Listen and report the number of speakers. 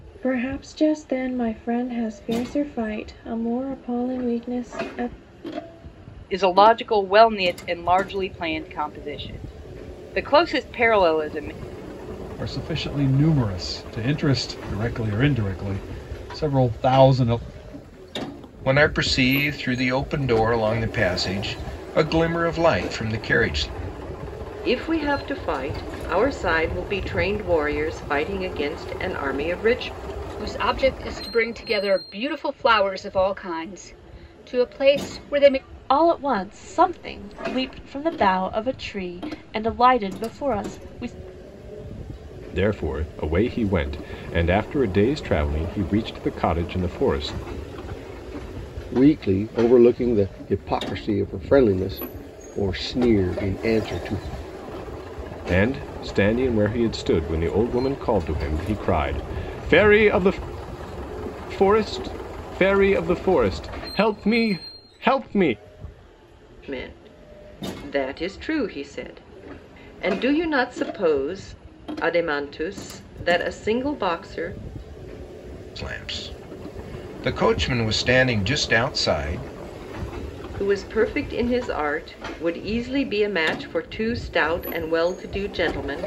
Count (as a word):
nine